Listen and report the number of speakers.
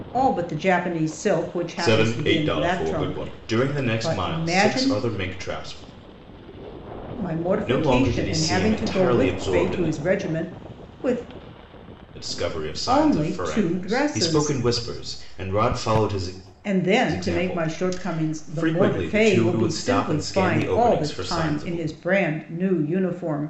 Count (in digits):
2